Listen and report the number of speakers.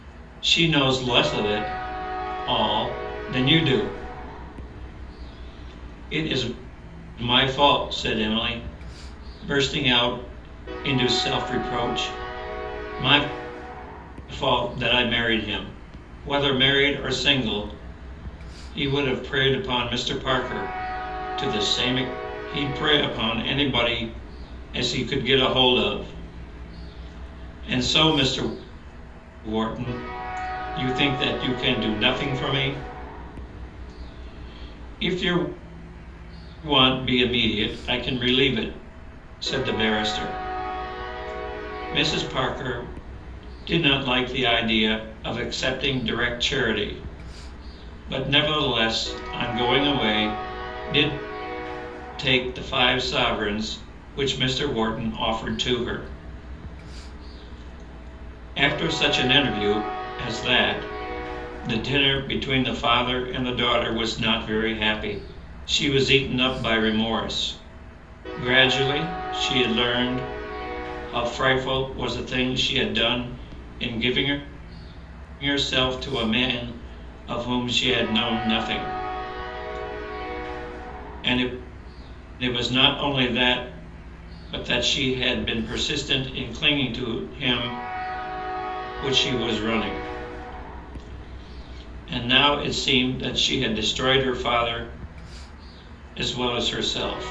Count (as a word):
one